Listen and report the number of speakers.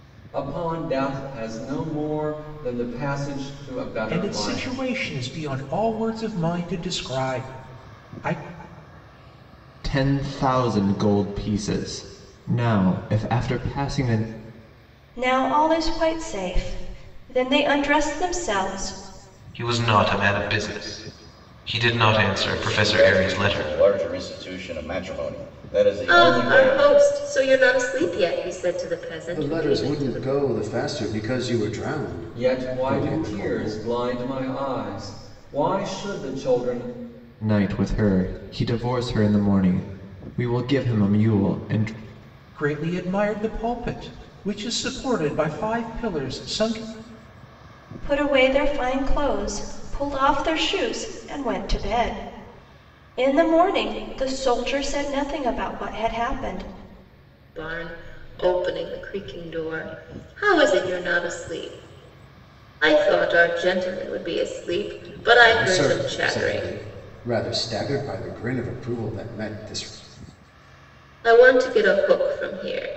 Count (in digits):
8